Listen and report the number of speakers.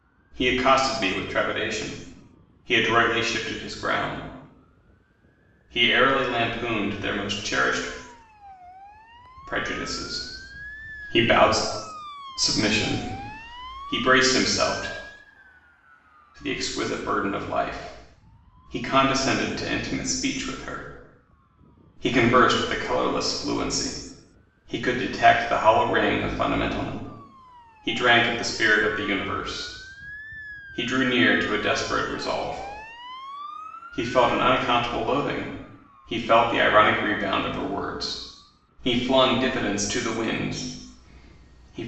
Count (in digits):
1